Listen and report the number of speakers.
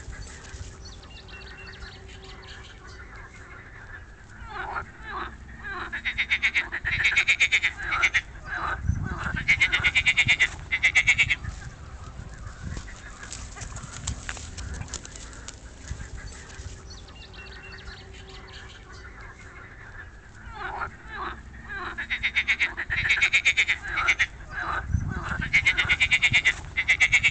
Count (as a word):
zero